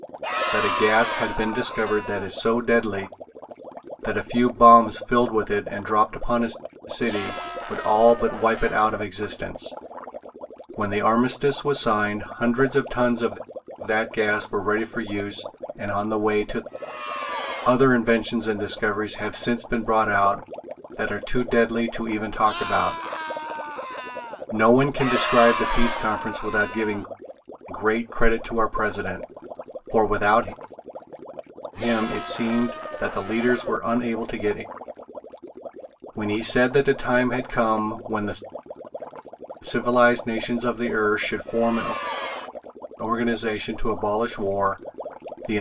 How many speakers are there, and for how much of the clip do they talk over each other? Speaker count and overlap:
1, no overlap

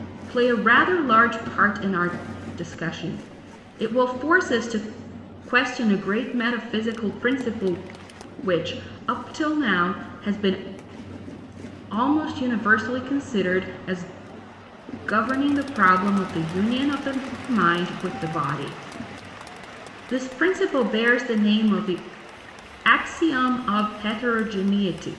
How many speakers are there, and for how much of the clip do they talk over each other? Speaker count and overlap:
1, no overlap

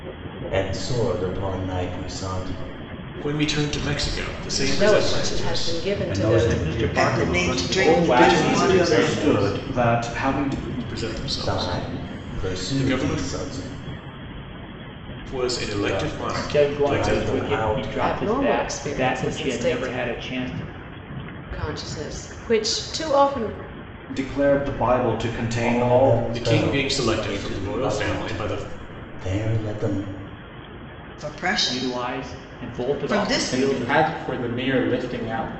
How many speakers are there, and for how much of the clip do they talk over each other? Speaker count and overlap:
9, about 46%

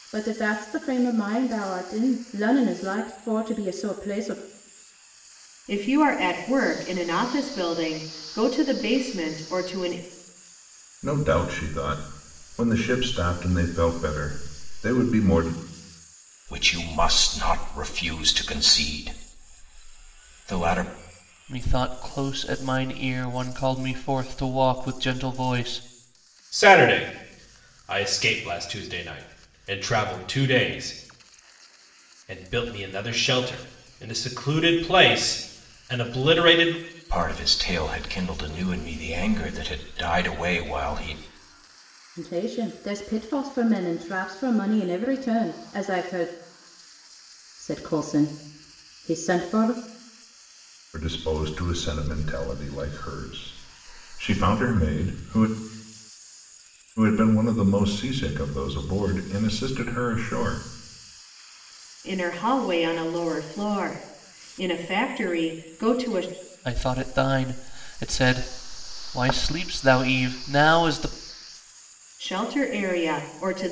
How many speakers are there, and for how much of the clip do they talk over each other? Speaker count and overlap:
6, no overlap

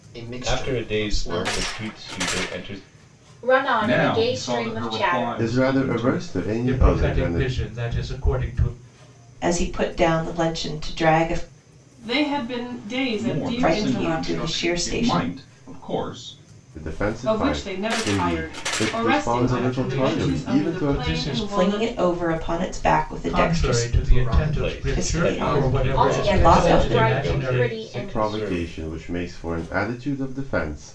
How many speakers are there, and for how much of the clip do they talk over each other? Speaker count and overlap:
8, about 55%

